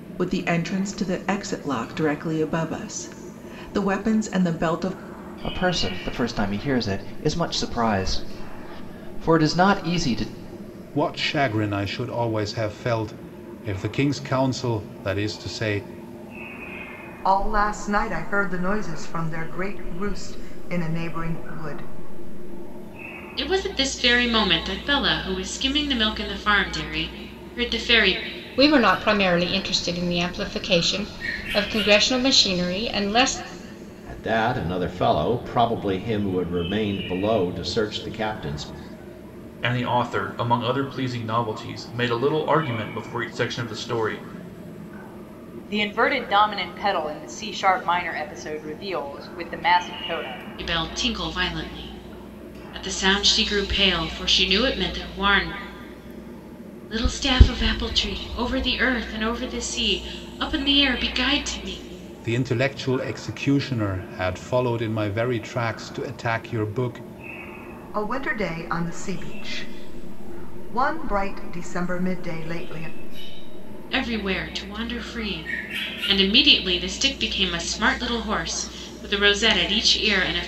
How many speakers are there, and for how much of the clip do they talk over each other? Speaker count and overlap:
nine, no overlap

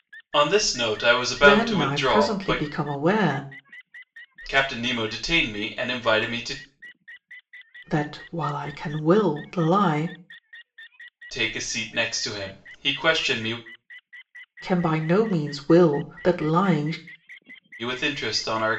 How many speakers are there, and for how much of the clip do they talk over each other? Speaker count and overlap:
two, about 7%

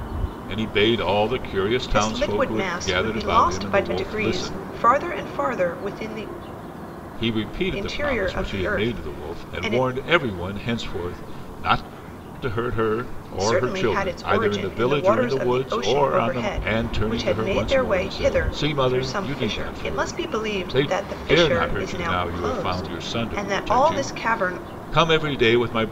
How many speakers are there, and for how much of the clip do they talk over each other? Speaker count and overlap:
two, about 61%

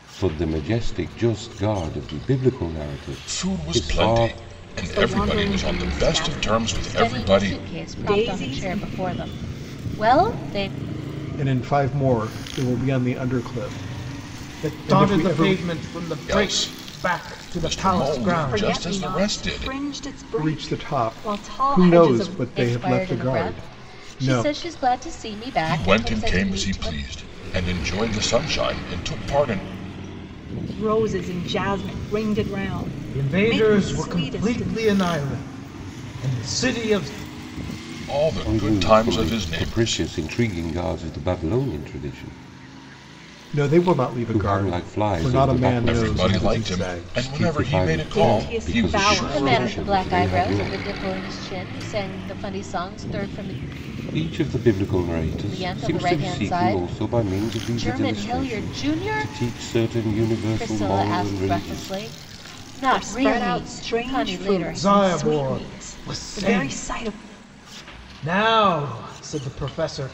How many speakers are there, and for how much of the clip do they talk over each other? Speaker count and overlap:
six, about 49%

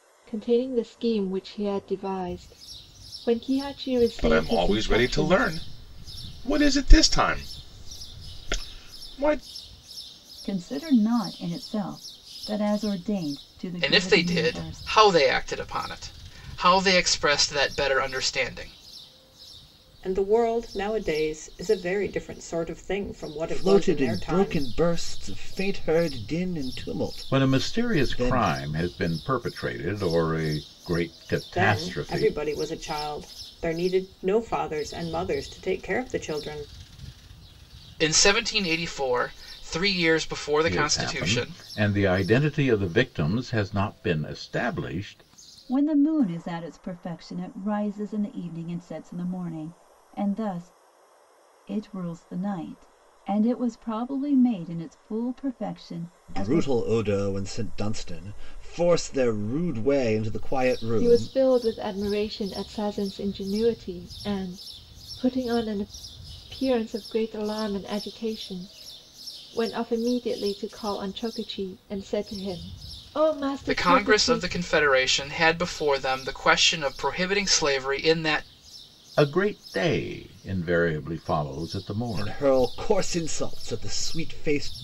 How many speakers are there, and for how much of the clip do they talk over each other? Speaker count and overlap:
seven, about 10%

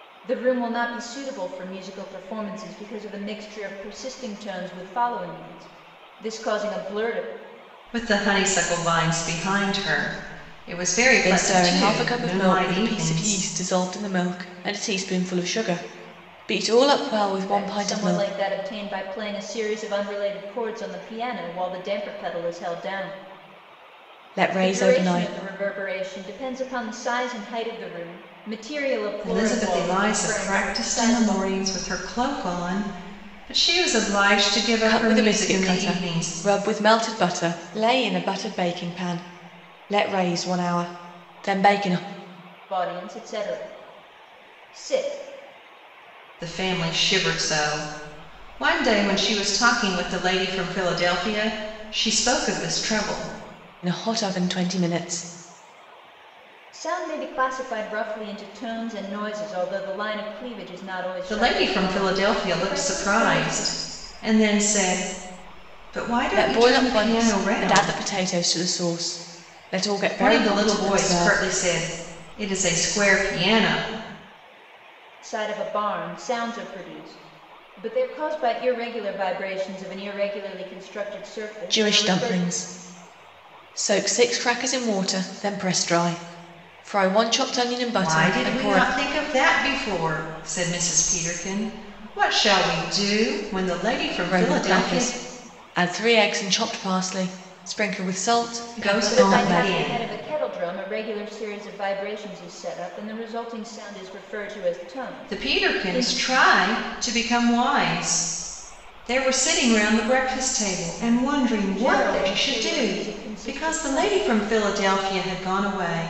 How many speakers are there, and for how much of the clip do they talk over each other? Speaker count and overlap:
three, about 18%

